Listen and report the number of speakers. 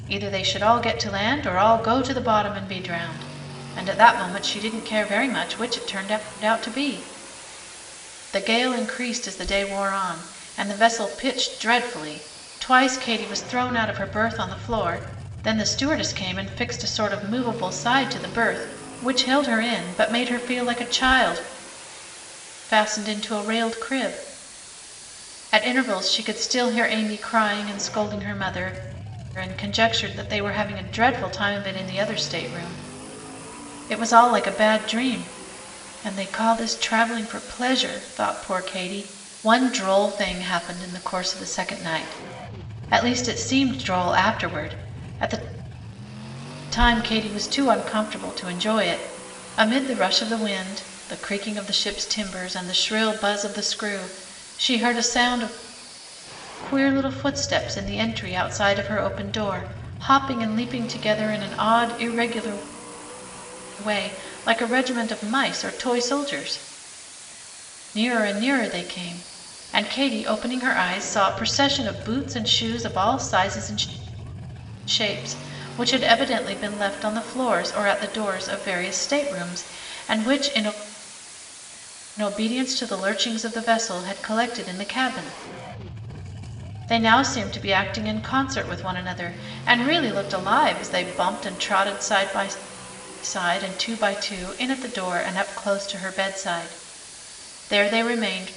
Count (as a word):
one